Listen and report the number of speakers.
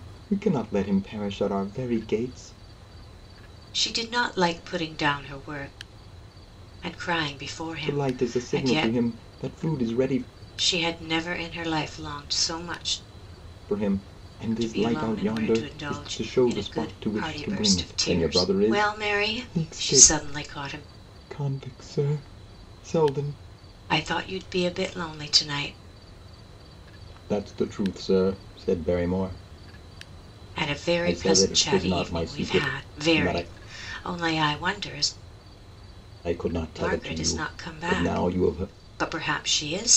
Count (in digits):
2